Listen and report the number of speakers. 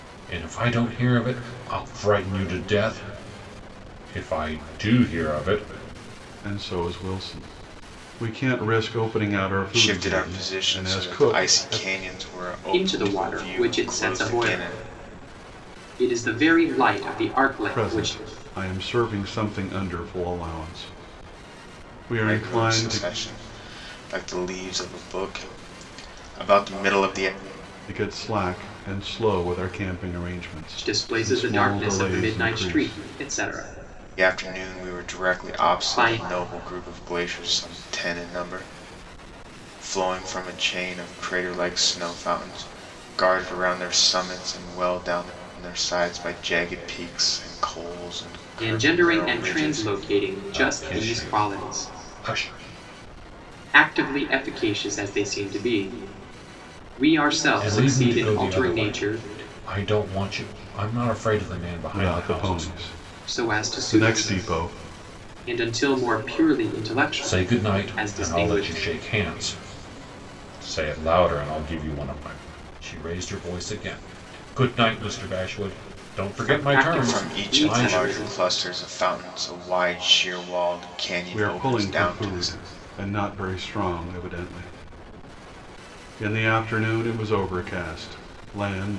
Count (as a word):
four